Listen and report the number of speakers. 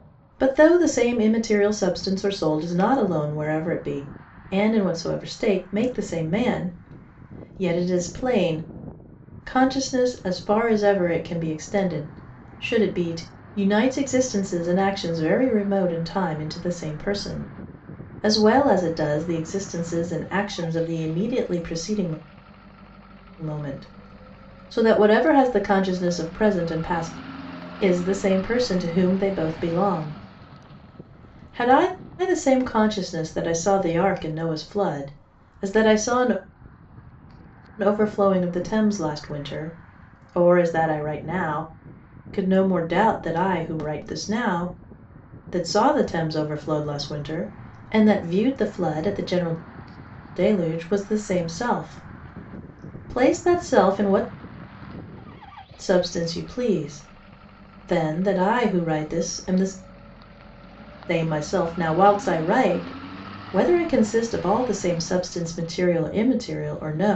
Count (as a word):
one